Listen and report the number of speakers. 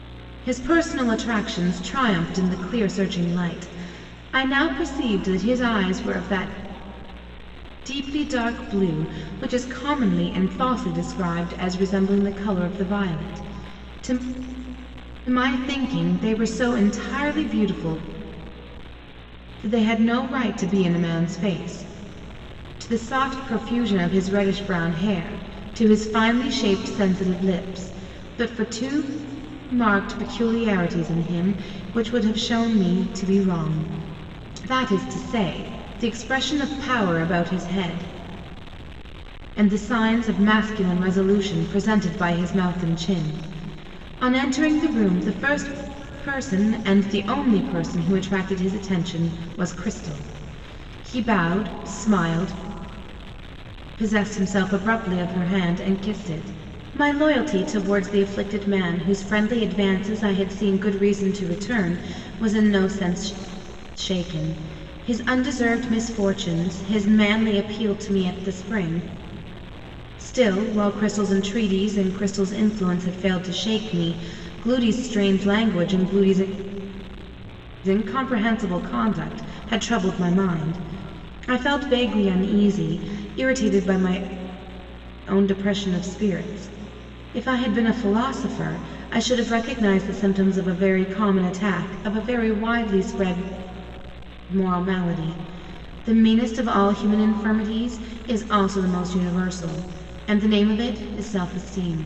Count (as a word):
one